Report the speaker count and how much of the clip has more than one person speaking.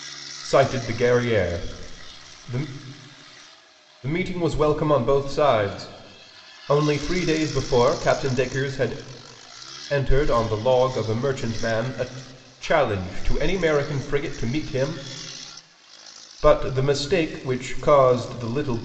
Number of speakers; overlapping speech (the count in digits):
1, no overlap